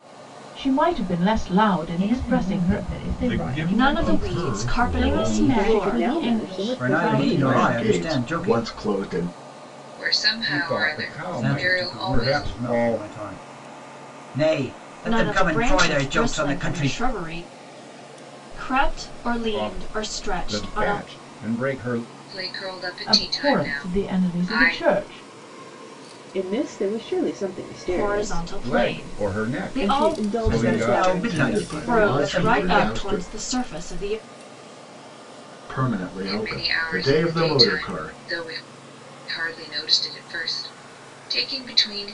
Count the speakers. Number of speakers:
10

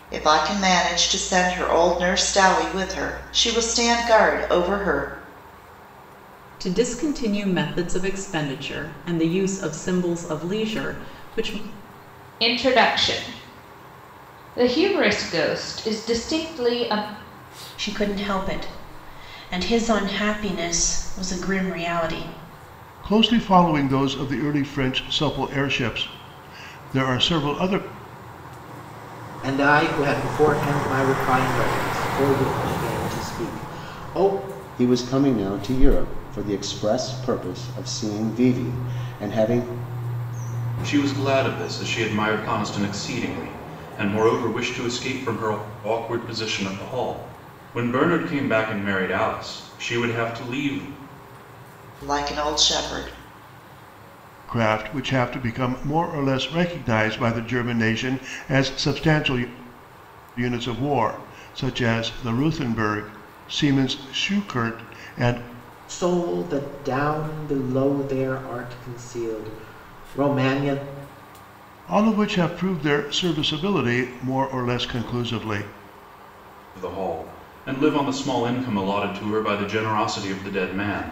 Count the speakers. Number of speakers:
8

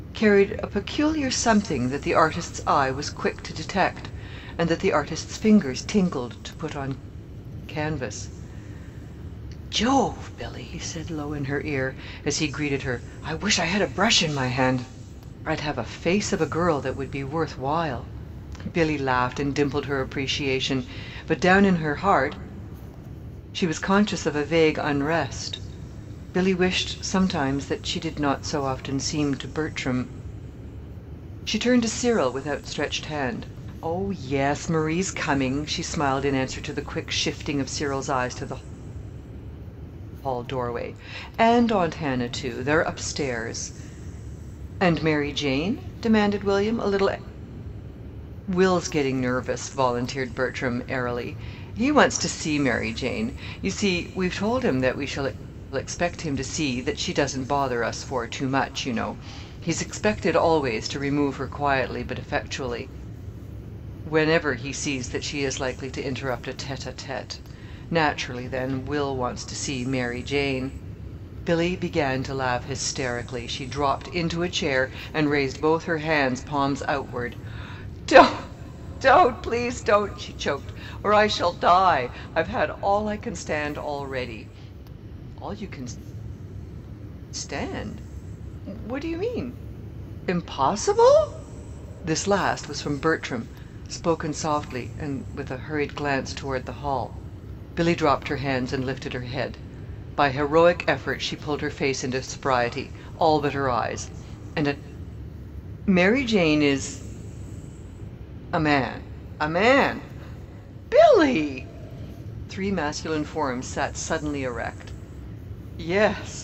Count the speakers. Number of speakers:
1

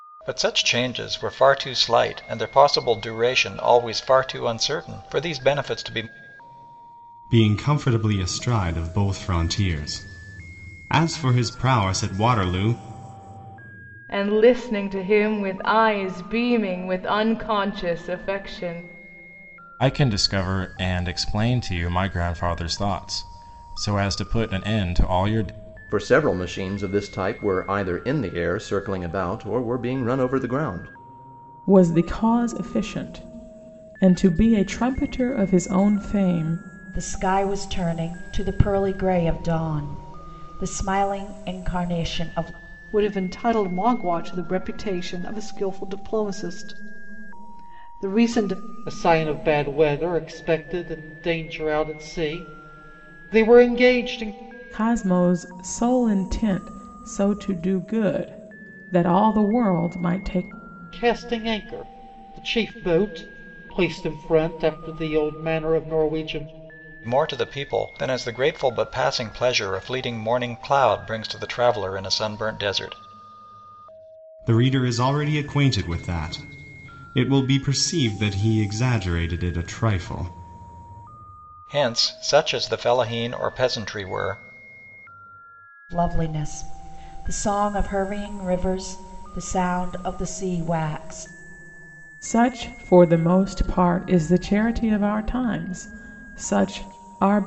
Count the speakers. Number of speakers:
9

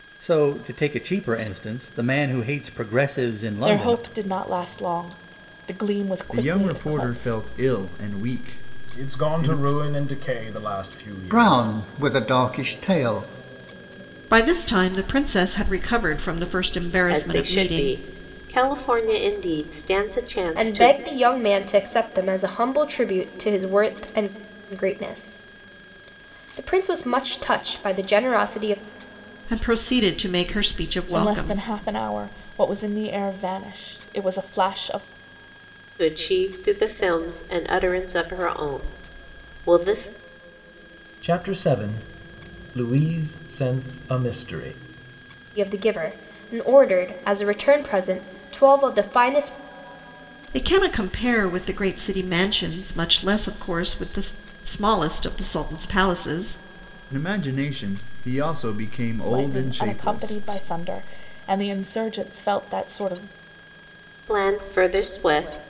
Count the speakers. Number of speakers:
8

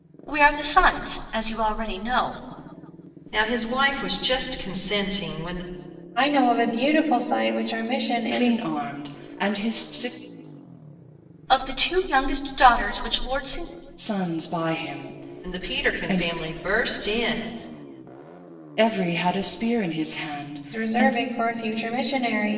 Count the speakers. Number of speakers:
4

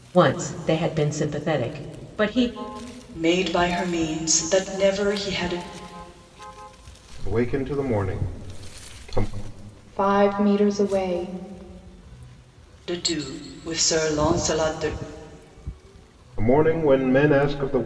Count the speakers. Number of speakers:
4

